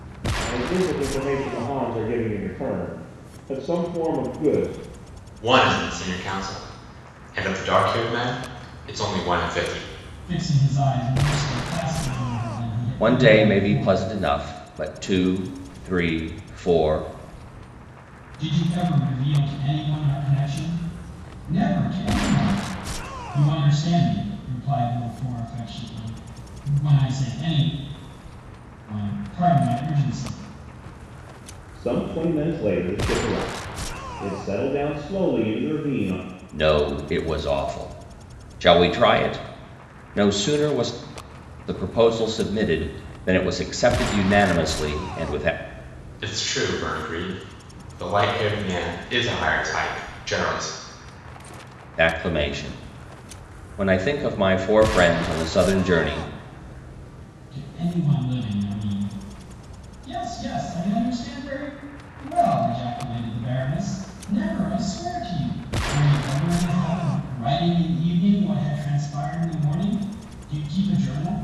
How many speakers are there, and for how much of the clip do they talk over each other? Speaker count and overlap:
4, about 1%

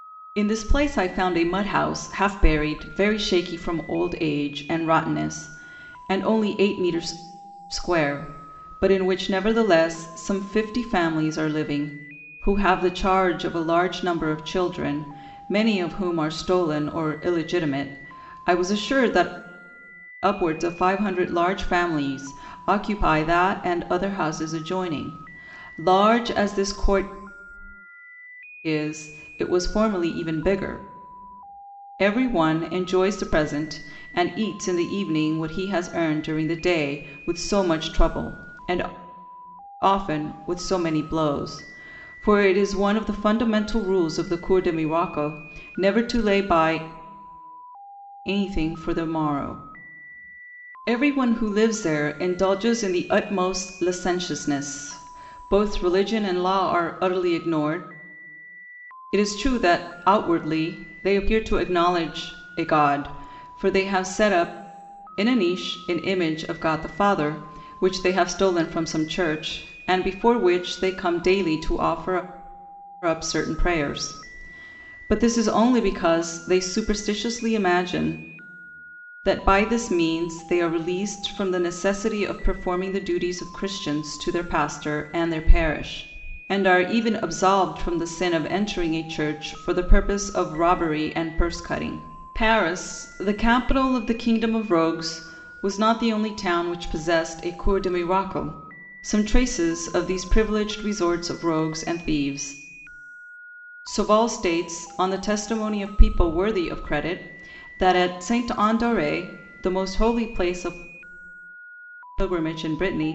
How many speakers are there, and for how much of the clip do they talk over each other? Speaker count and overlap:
1, no overlap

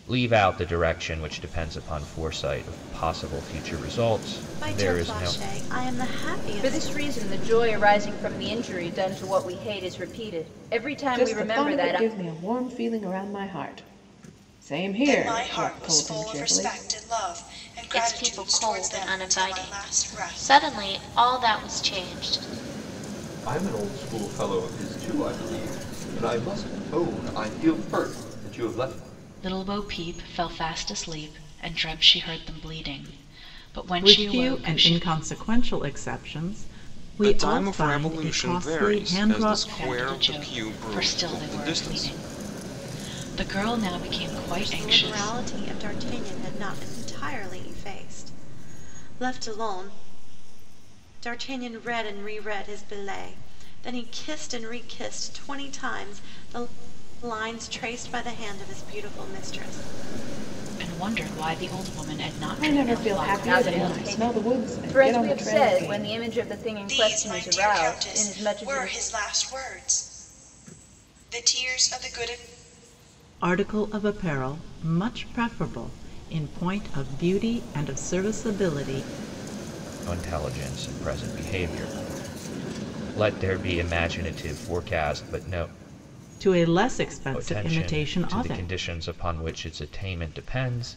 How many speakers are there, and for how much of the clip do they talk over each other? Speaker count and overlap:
10, about 23%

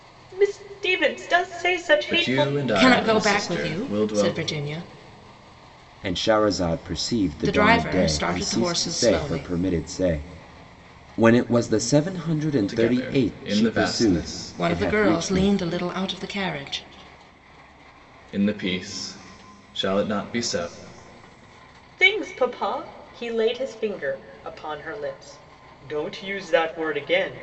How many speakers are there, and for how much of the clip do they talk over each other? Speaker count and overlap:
4, about 27%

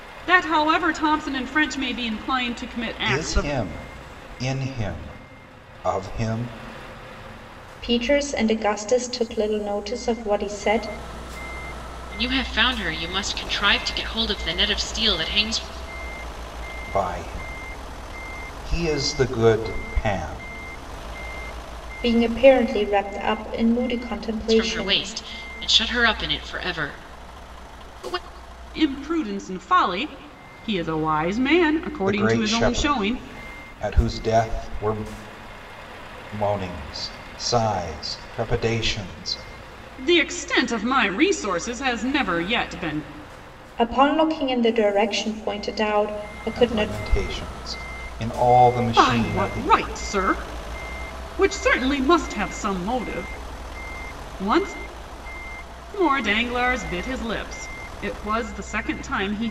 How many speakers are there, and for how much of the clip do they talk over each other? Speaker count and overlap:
4, about 6%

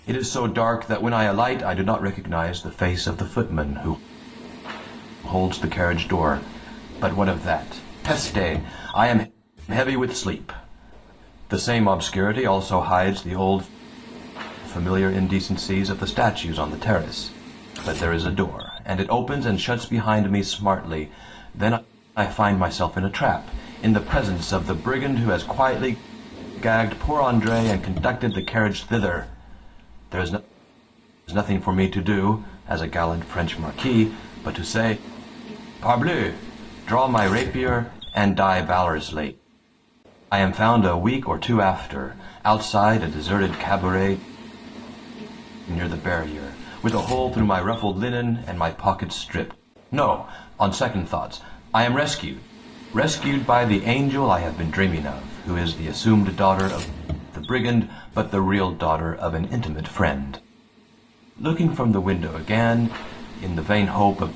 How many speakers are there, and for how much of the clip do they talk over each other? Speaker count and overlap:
1, no overlap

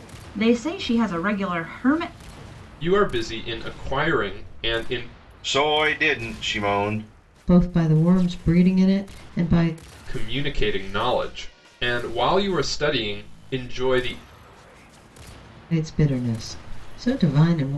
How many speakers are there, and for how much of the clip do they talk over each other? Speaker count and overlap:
4, no overlap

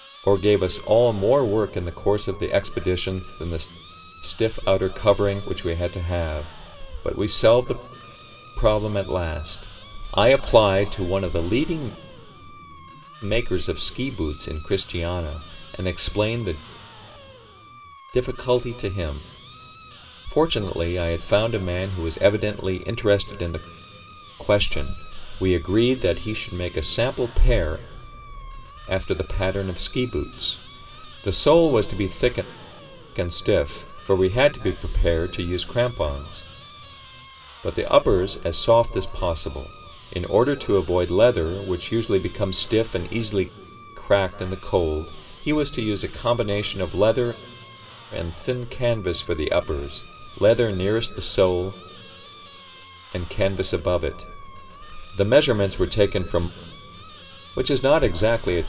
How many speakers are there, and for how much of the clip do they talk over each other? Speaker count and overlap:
1, no overlap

